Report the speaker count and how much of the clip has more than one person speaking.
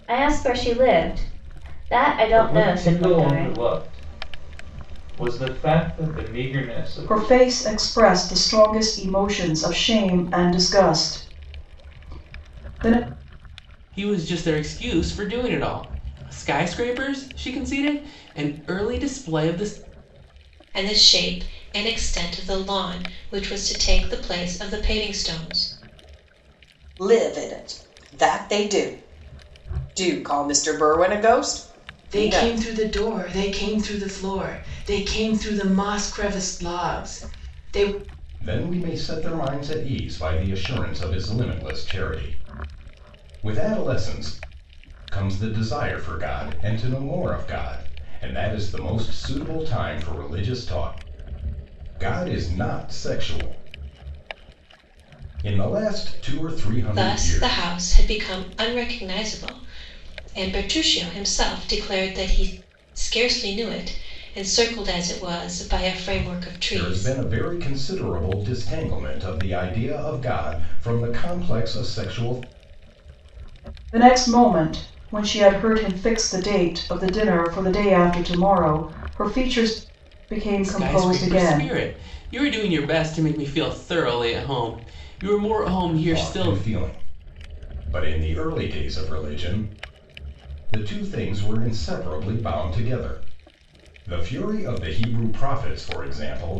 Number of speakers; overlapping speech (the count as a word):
eight, about 5%